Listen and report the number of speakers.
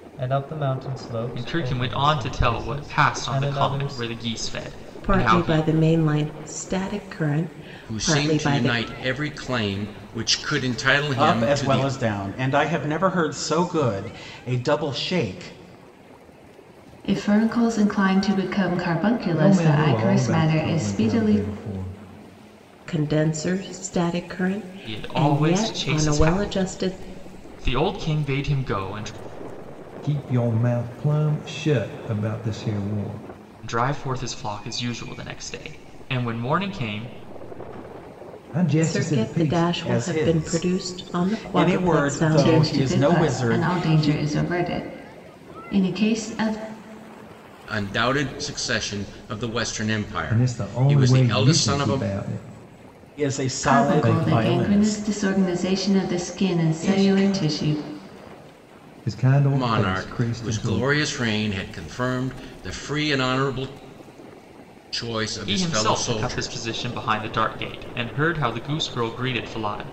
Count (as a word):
seven